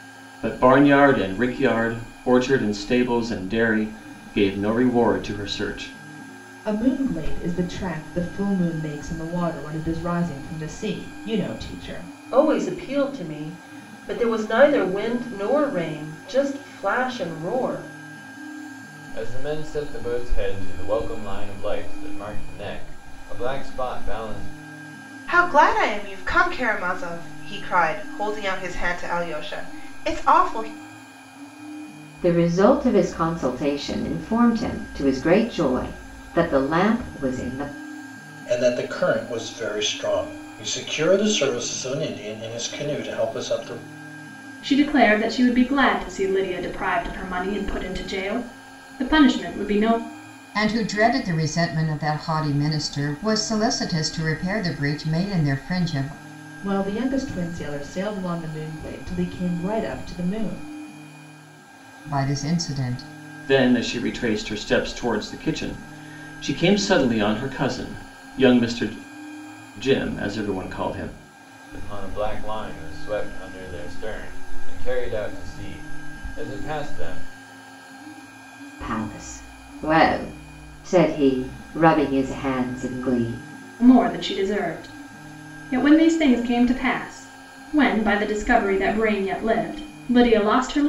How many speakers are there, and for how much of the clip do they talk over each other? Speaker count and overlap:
nine, no overlap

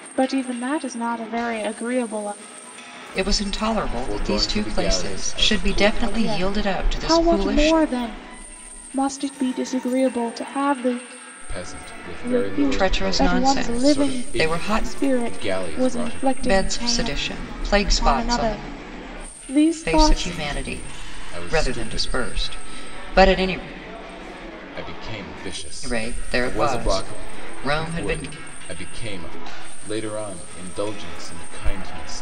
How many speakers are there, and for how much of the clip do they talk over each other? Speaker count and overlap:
three, about 41%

